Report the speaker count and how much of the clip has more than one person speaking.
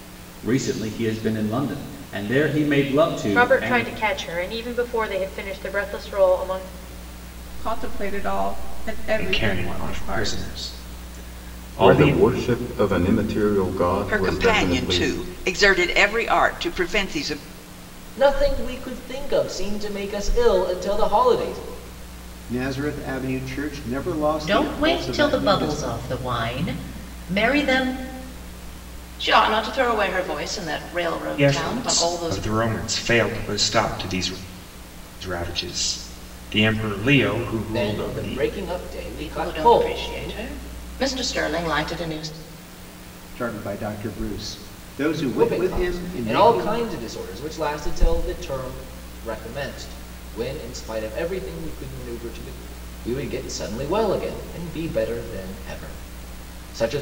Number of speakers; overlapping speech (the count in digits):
10, about 18%